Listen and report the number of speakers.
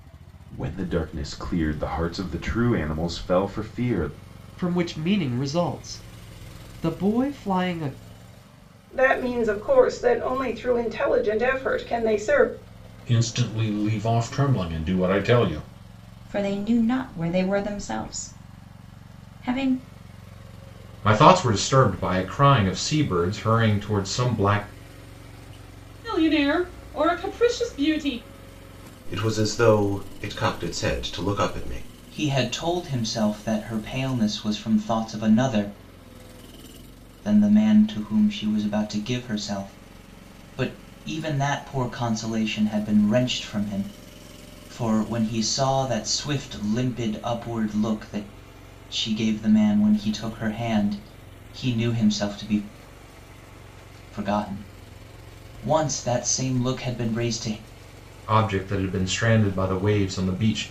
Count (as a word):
nine